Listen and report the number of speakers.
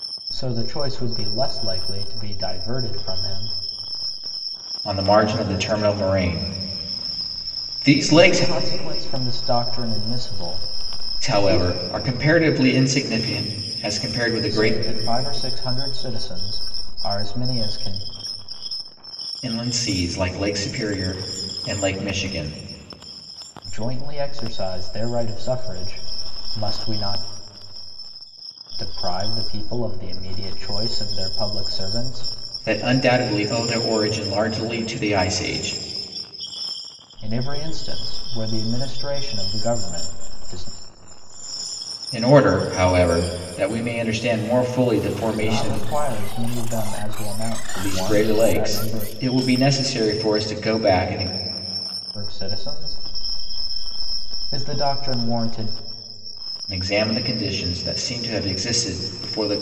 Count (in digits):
2